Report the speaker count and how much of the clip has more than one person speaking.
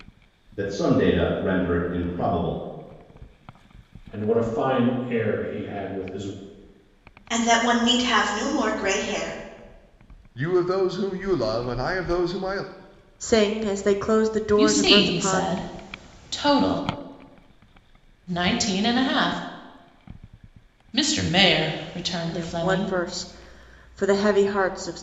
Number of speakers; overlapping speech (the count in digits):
6, about 7%